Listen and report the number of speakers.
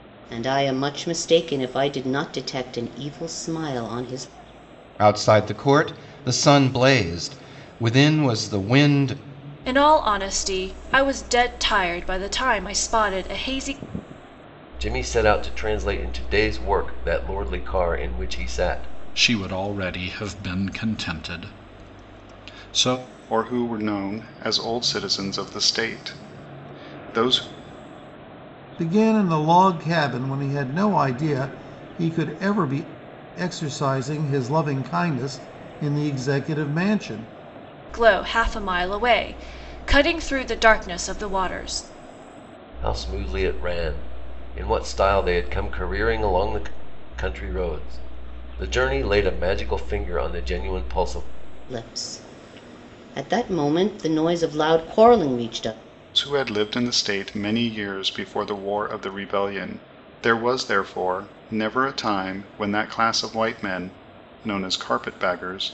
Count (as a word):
seven